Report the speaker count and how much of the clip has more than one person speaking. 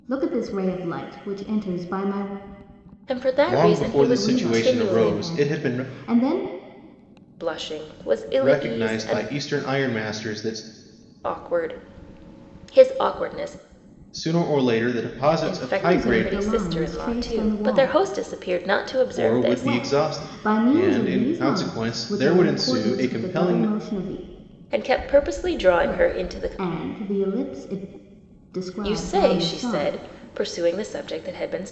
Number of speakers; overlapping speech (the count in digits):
3, about 39%